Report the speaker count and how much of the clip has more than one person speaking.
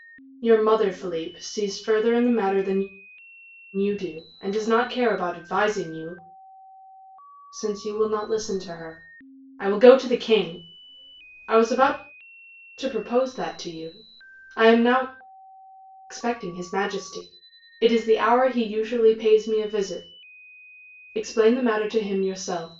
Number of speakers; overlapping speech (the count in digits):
1, no overlap